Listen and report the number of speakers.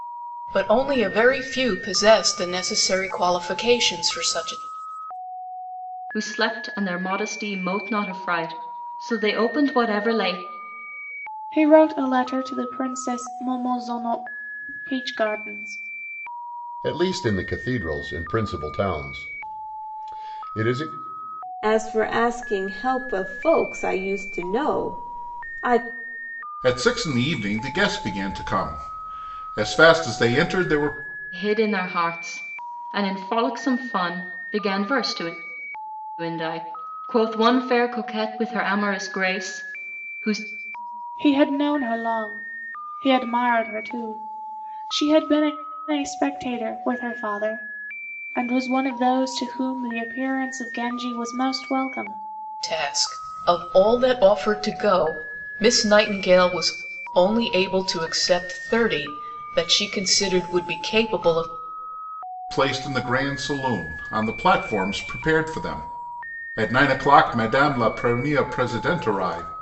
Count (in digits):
6